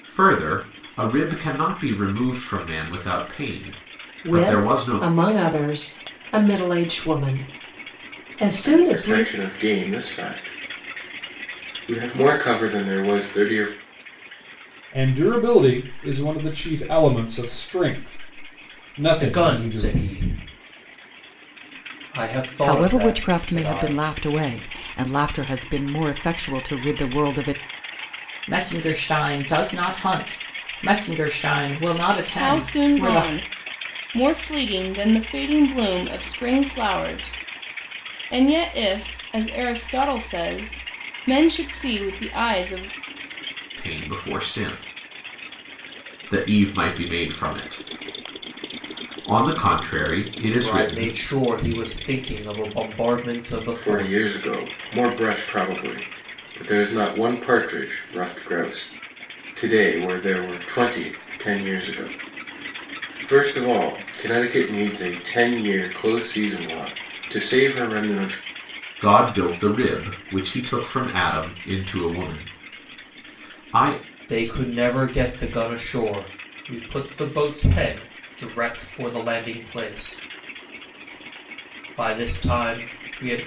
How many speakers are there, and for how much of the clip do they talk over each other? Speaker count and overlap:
eight, about 7%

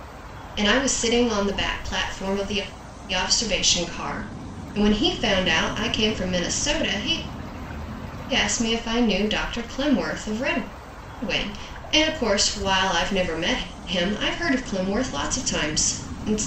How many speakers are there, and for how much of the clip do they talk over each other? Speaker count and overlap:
one, no overlap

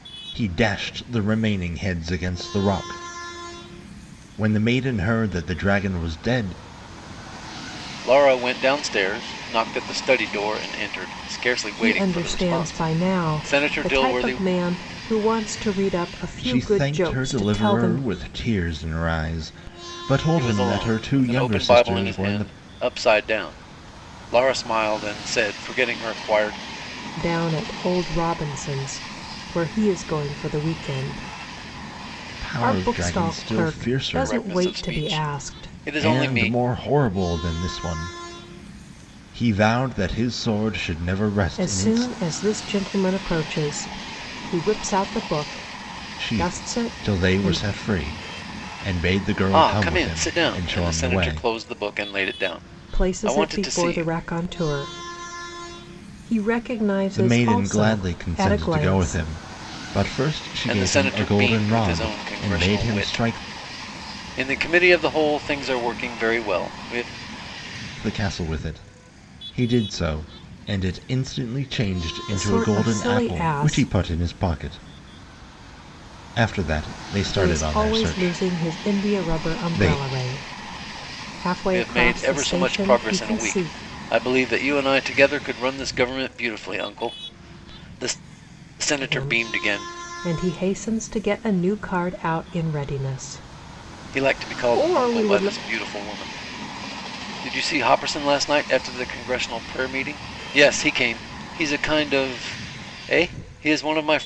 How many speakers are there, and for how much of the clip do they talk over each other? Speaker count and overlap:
three, about 28%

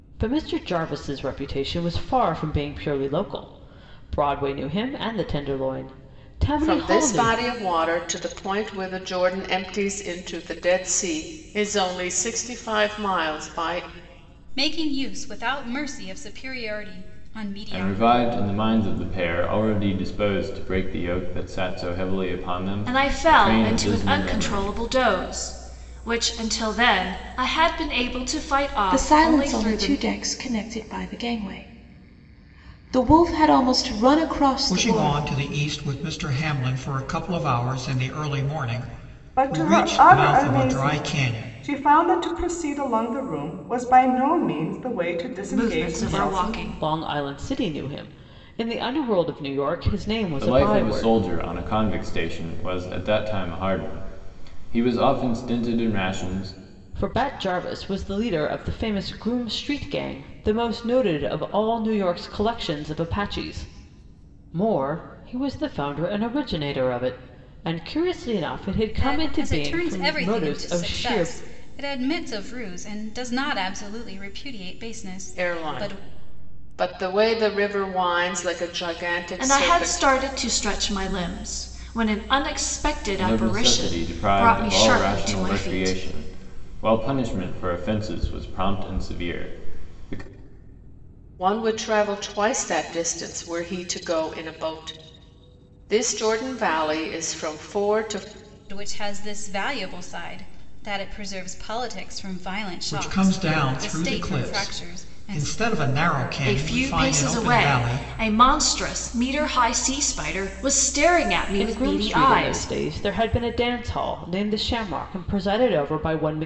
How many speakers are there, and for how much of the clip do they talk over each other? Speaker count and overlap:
eight, about 19%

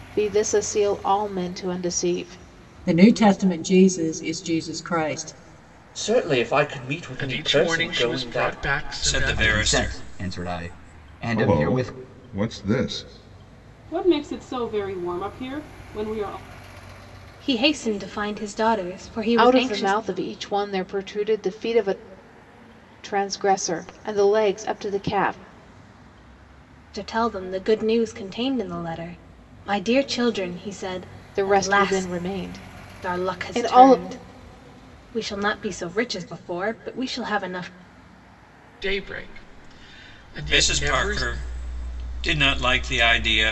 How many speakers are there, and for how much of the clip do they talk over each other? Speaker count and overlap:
nine, about 15%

